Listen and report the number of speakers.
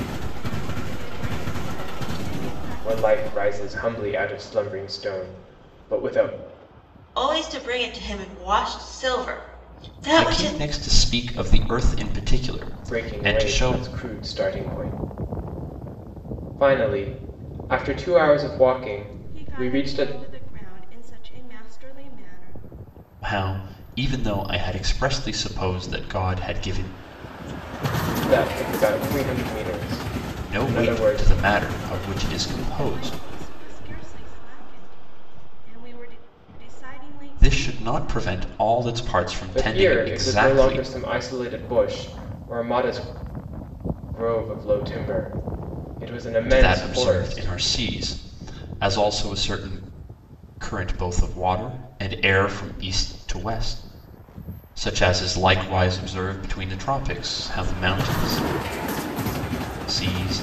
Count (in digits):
4